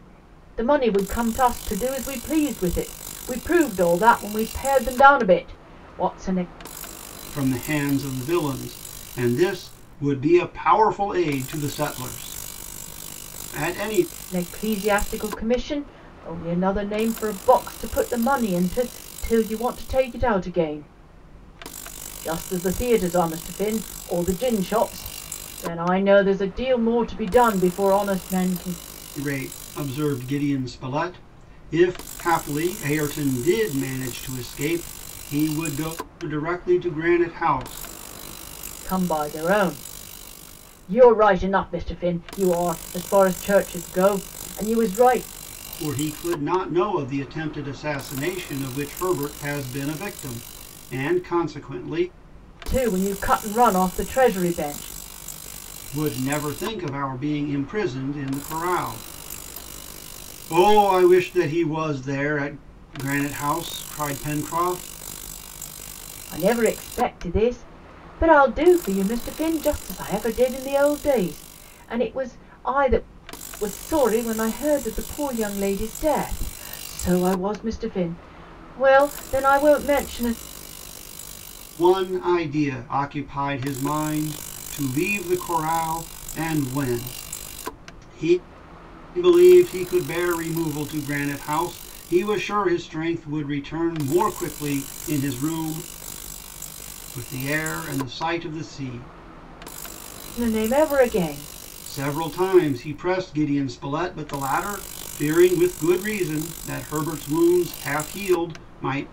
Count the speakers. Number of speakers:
2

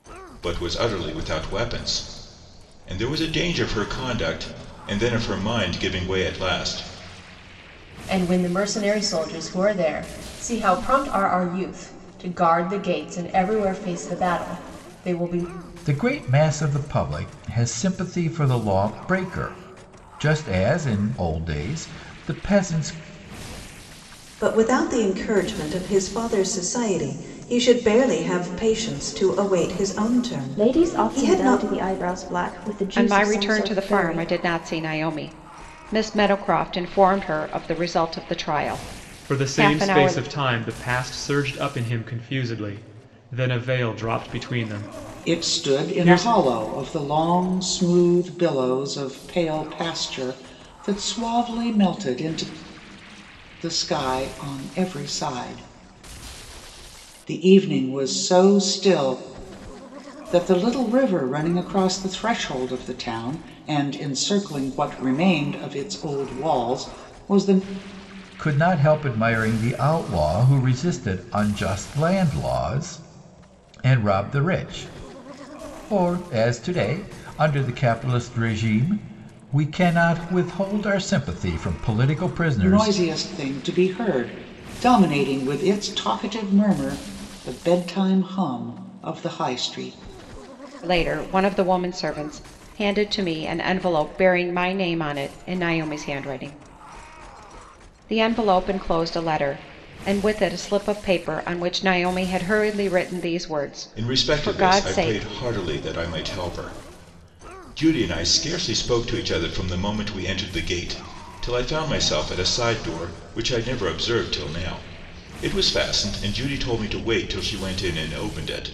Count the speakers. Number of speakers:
8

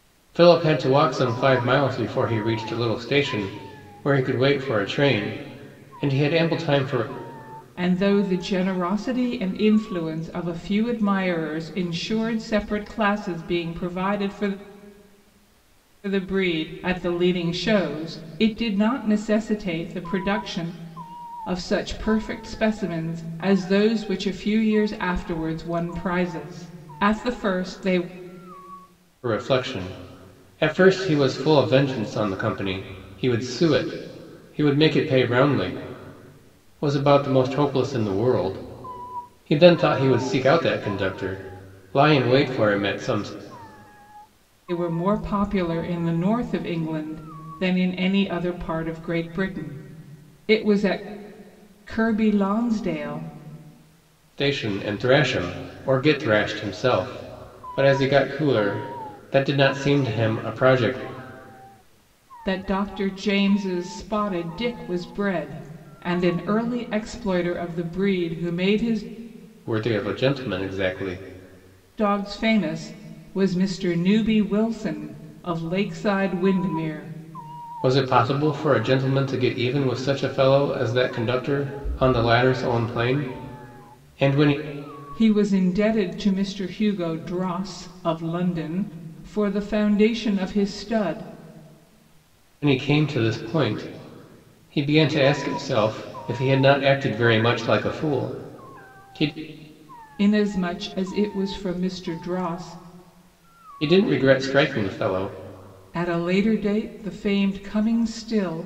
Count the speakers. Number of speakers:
2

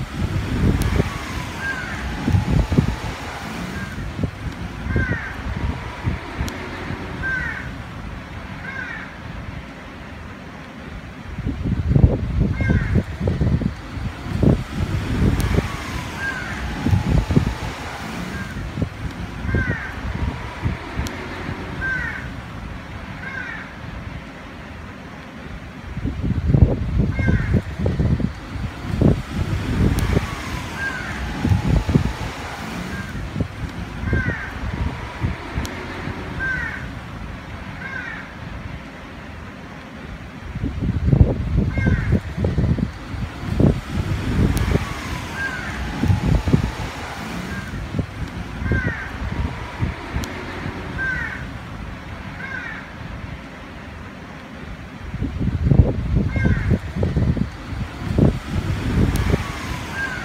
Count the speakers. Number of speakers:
0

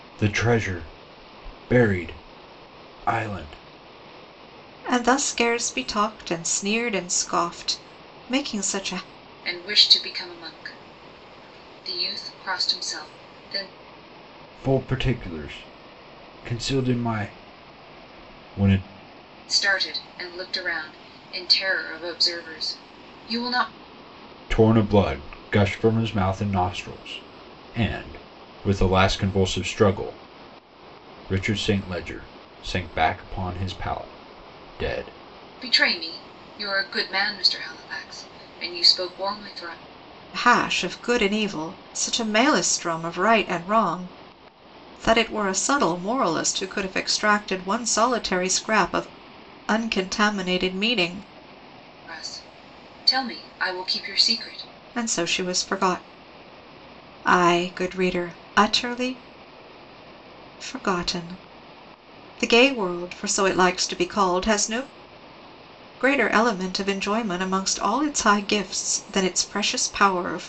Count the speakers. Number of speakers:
3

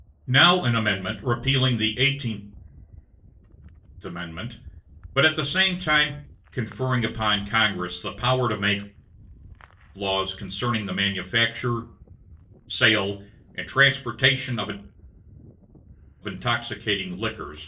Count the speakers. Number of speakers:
1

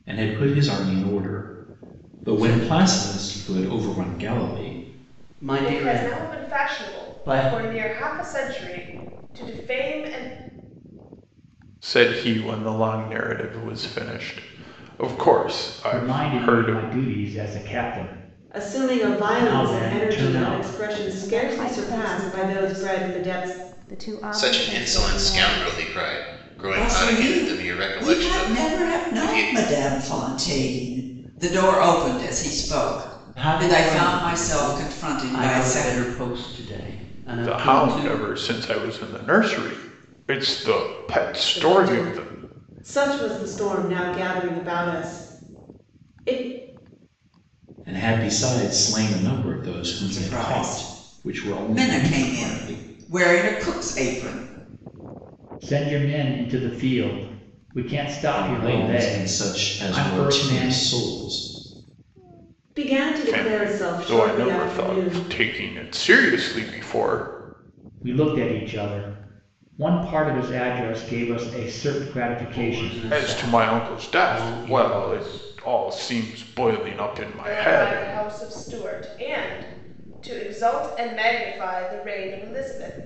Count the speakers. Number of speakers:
9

